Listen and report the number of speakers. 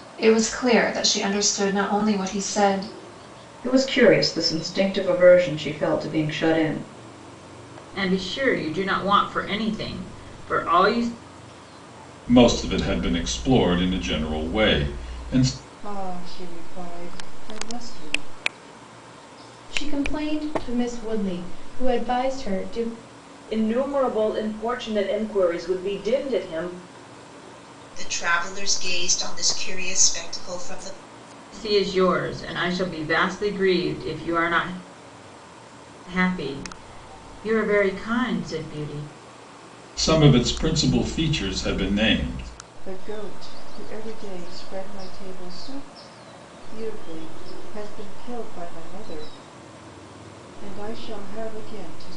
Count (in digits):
8